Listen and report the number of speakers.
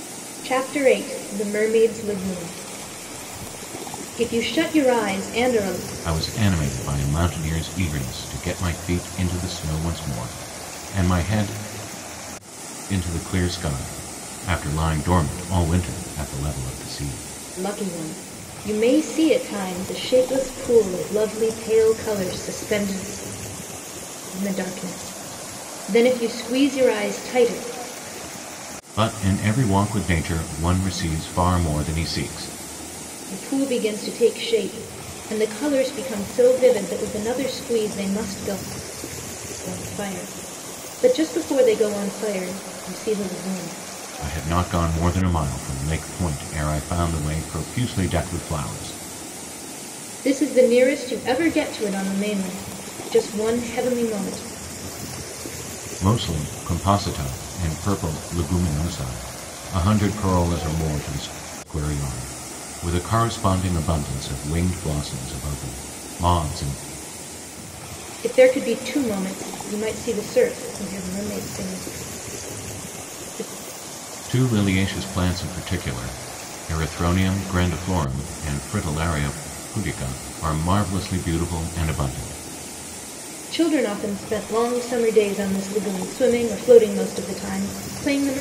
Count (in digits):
2